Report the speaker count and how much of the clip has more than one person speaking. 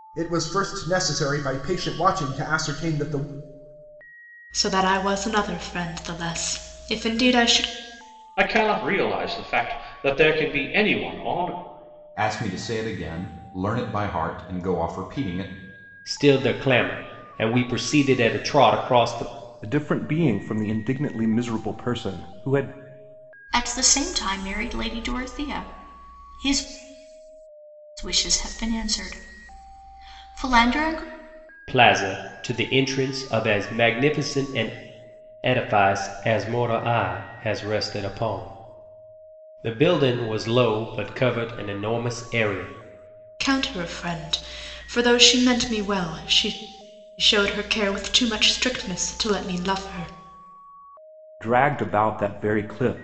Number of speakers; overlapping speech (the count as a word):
seven, no overlap